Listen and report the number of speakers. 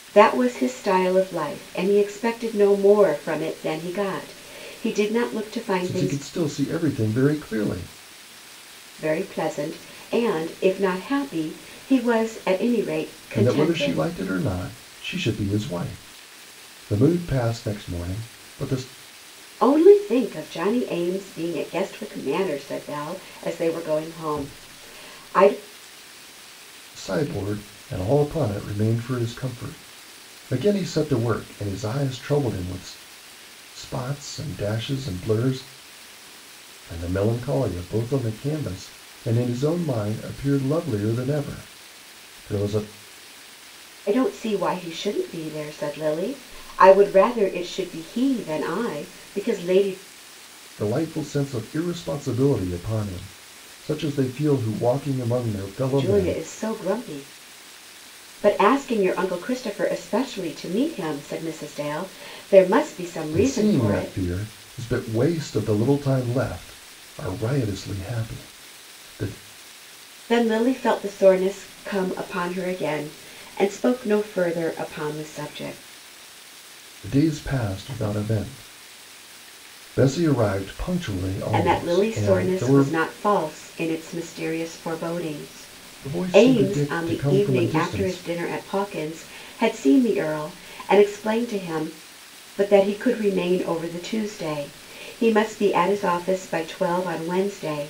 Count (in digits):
2